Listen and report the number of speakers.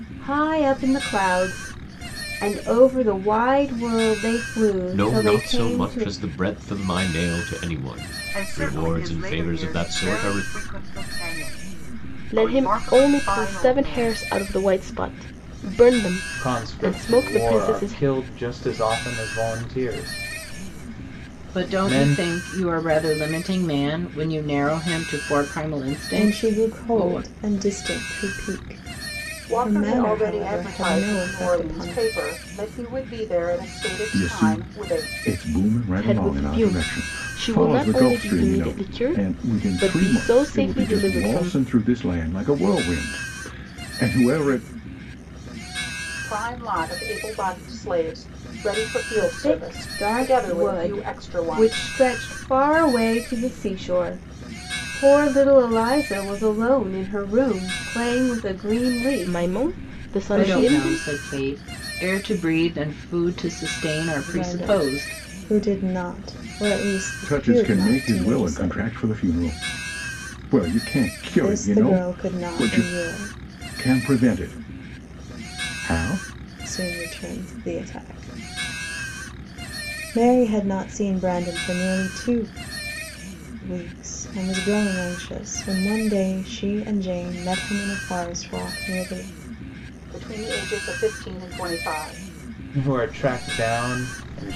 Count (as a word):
nine